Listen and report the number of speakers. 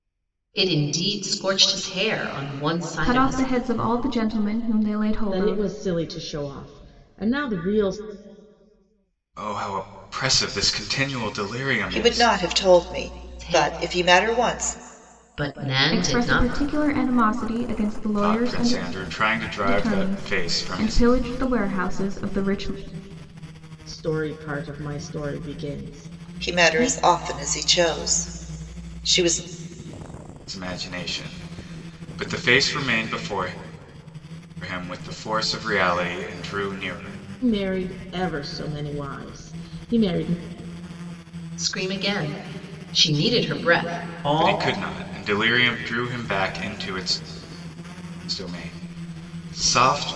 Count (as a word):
five